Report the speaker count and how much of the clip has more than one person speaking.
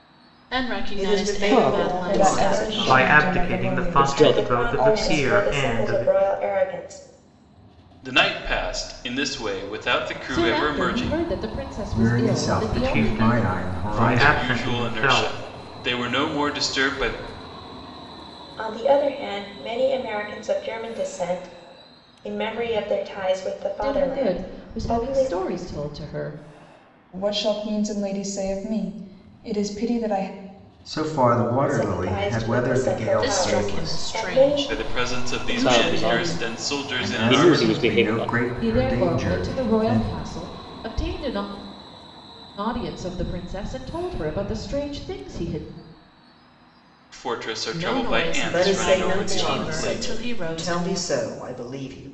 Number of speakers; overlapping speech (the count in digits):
9, about 43%